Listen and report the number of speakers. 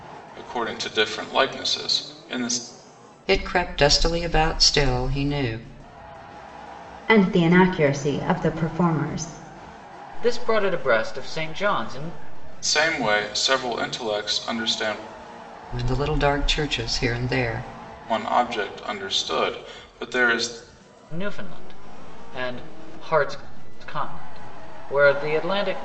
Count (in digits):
4